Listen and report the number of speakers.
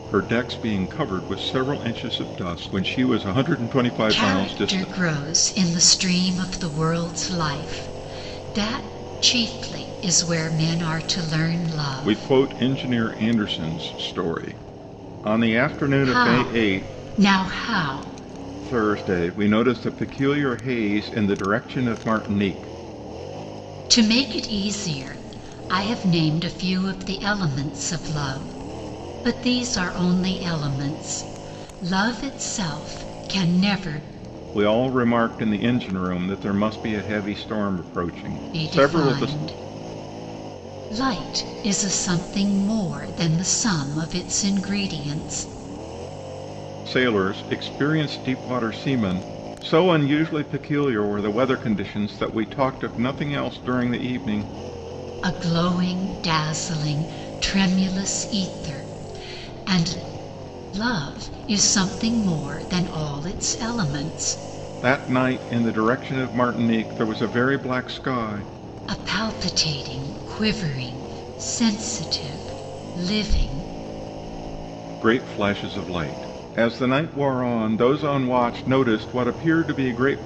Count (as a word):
two